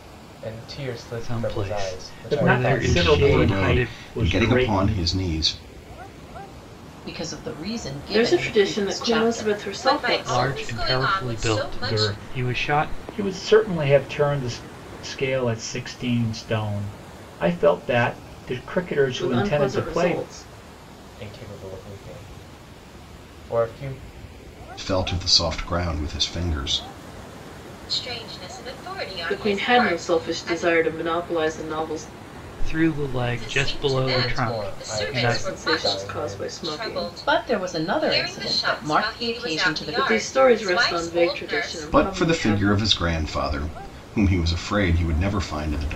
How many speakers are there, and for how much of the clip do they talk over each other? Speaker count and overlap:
seven, about 44%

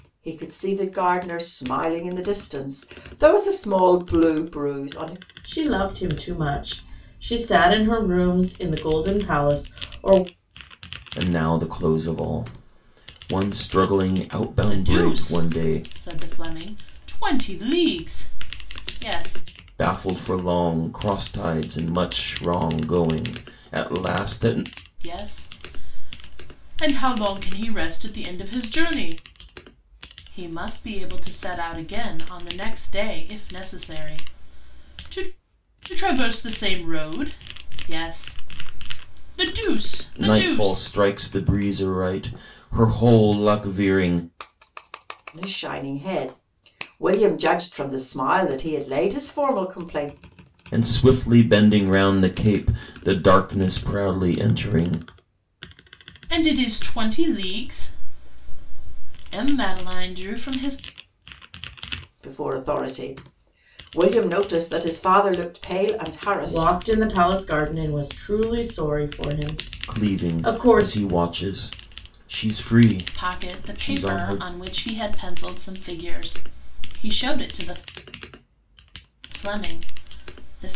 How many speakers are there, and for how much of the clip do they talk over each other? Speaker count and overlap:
four, about 6%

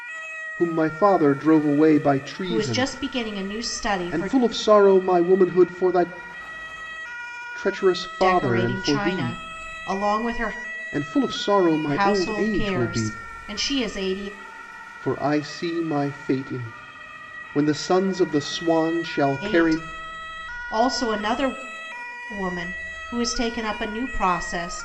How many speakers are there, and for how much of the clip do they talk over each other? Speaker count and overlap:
two, about 15%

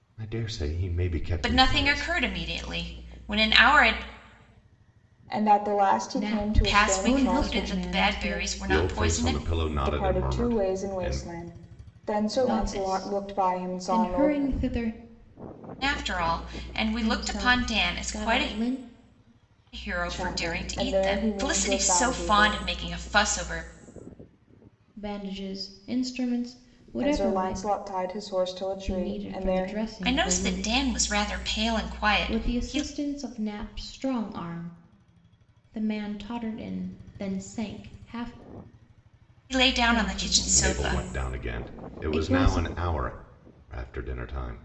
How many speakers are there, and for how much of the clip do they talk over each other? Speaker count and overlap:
four, about 39%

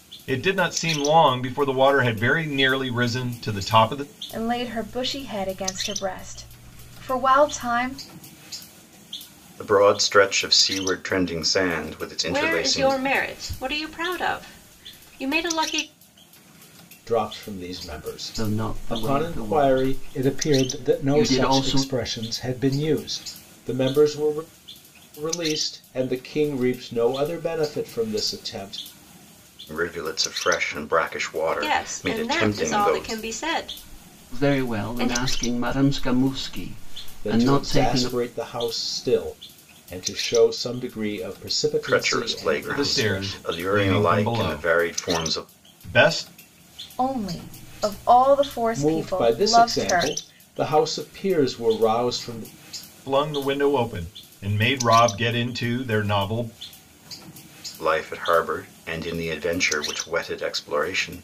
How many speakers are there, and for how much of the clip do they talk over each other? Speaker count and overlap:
six, about 21%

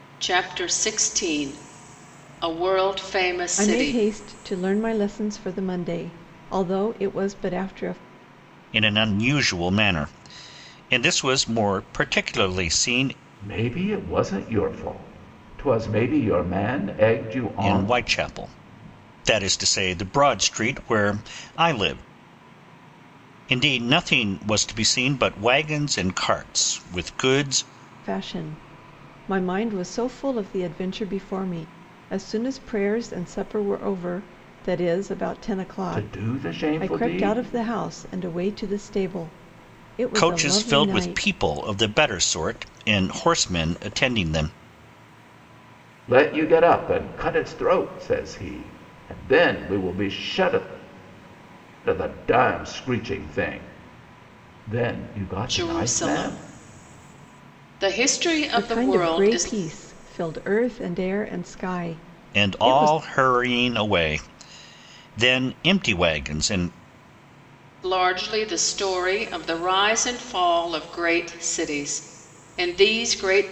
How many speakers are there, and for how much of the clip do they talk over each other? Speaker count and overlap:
four, about 8%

